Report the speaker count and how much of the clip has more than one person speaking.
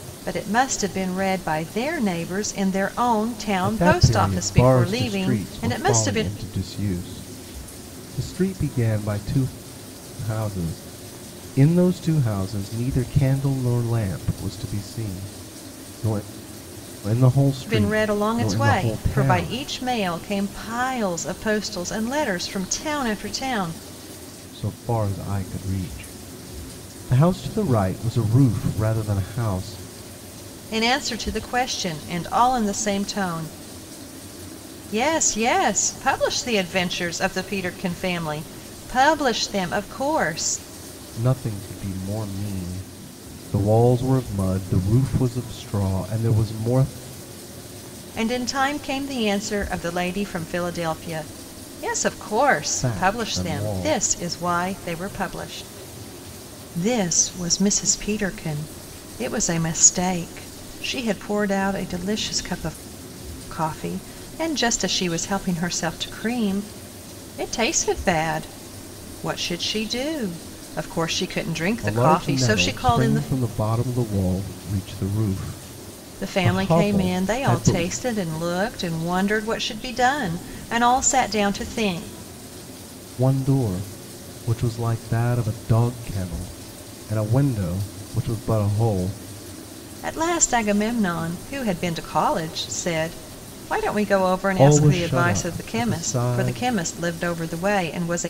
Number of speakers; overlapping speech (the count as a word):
two, about 12%